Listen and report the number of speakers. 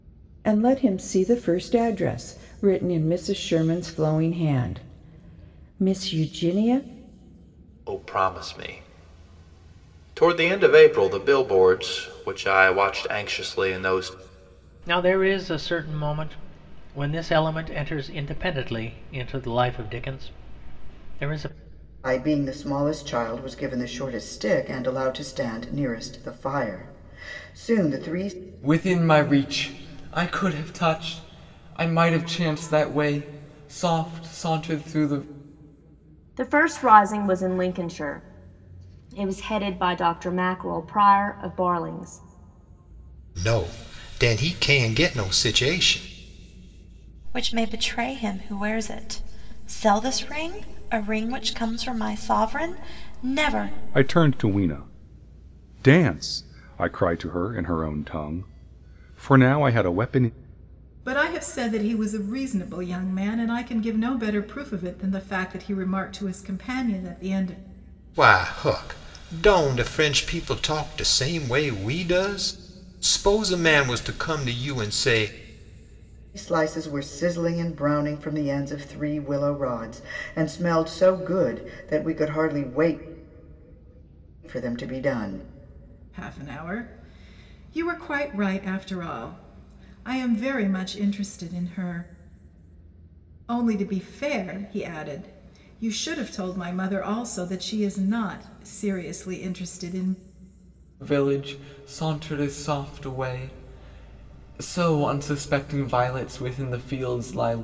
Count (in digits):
10